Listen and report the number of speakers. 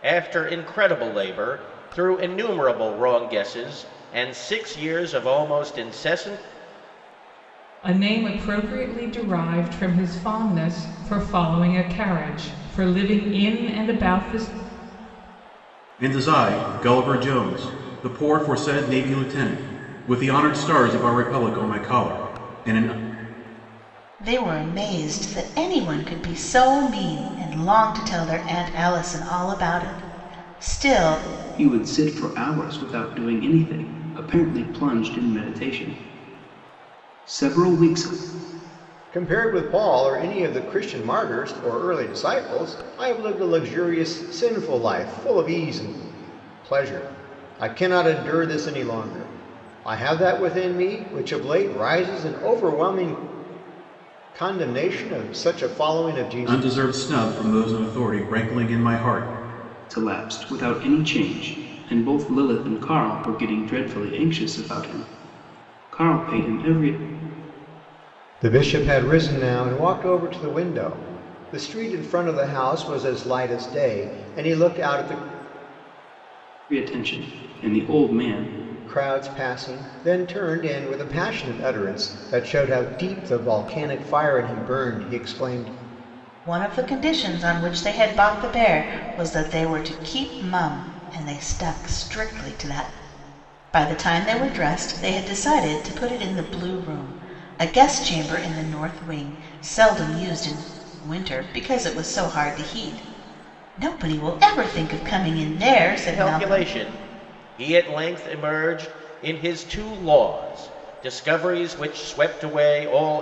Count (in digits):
6